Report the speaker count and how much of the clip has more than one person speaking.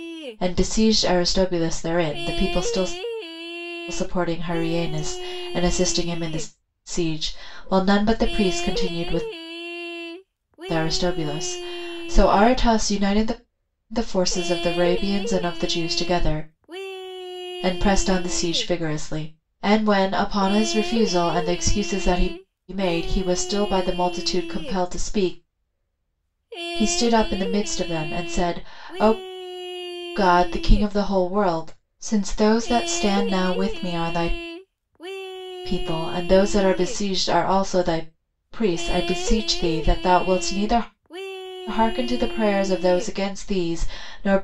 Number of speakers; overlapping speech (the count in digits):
1, no overlap